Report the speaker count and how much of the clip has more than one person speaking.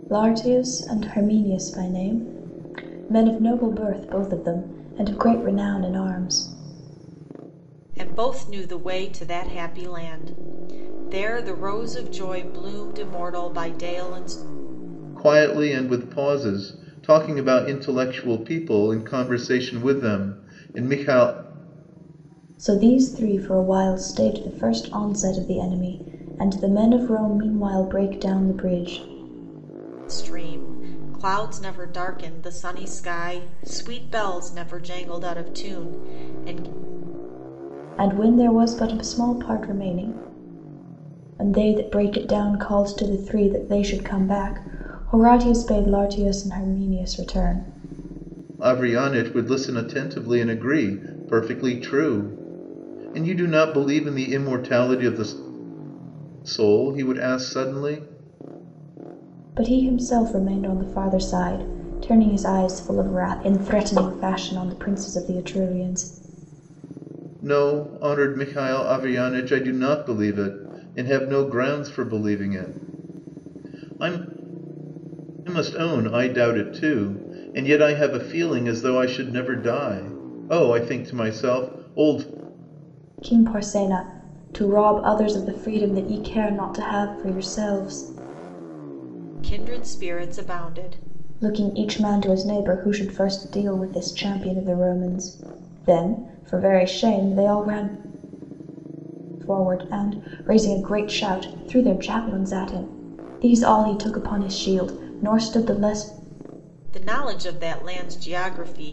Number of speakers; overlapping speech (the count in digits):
3, no overlap